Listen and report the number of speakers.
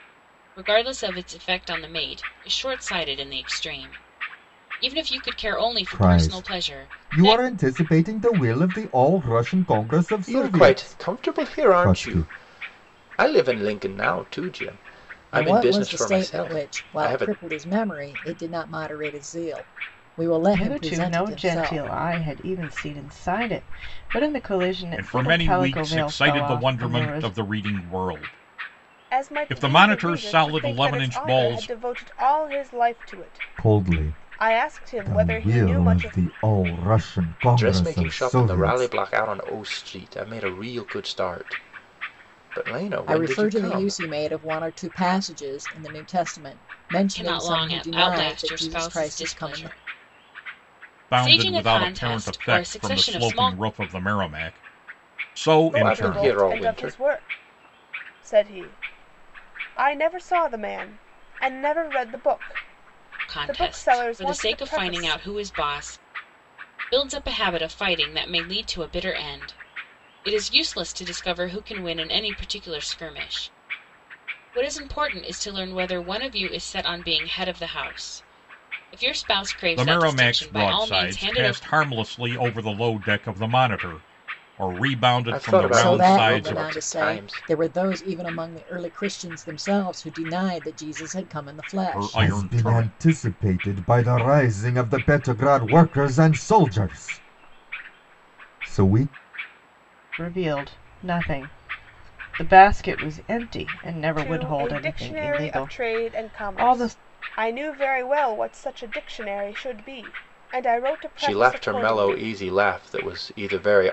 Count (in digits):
7